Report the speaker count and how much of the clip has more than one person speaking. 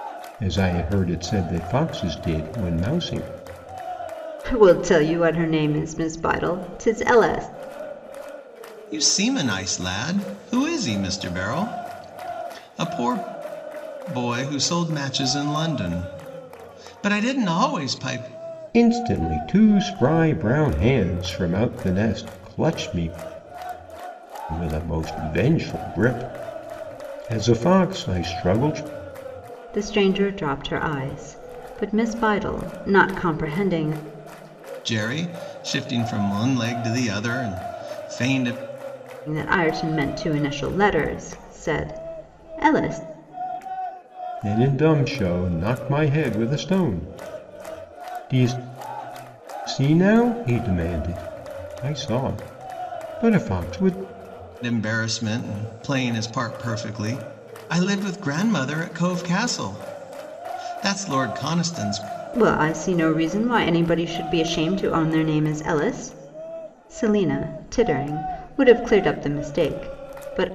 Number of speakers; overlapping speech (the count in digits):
3, no overlap